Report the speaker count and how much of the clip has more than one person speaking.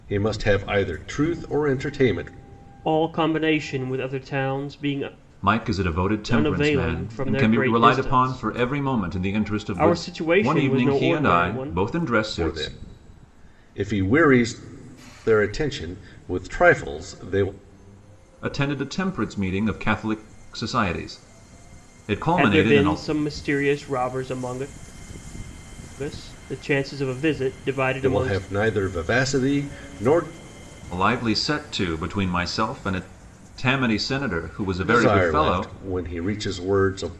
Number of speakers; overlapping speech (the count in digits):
3, about 17%